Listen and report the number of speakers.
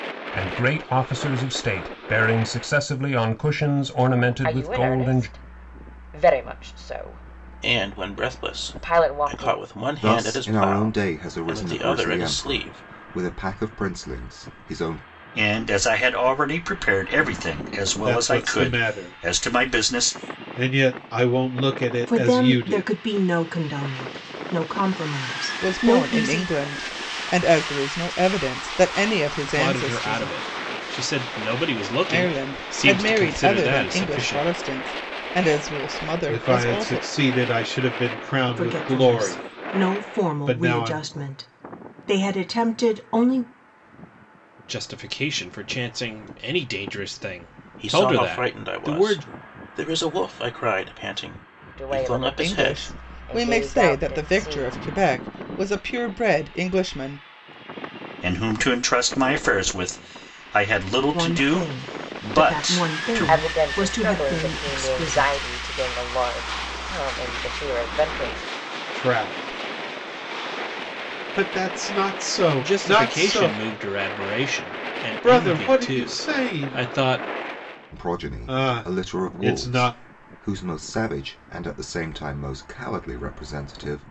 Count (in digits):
9